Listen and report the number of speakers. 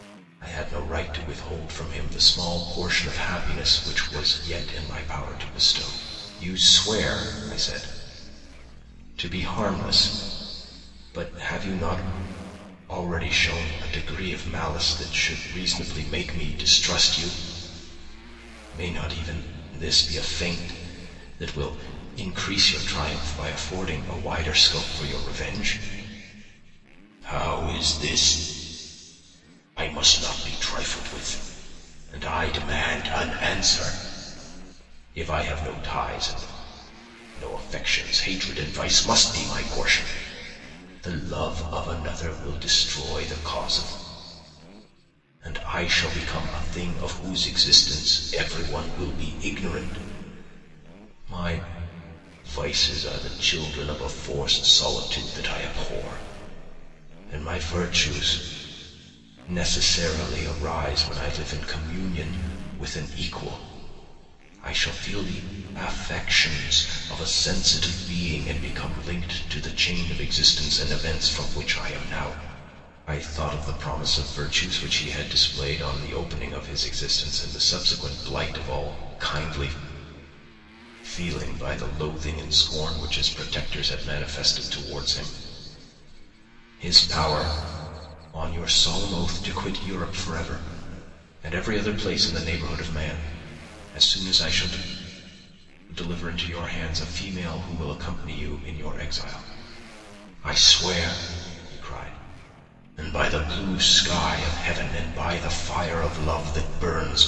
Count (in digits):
1